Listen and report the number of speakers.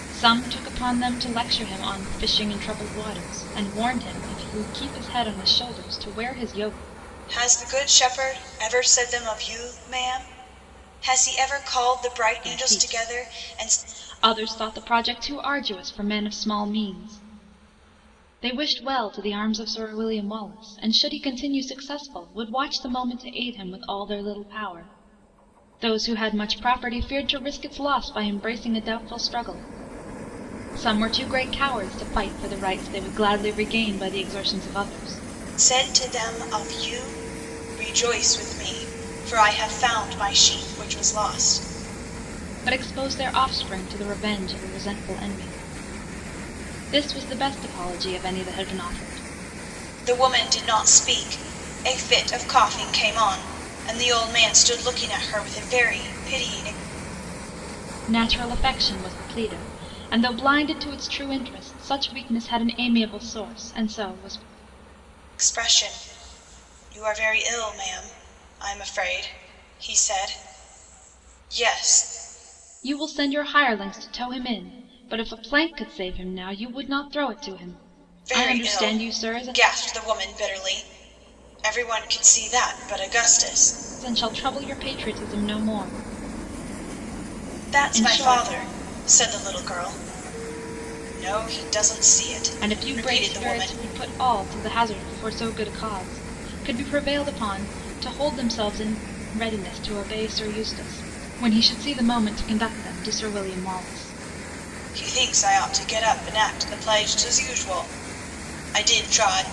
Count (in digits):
2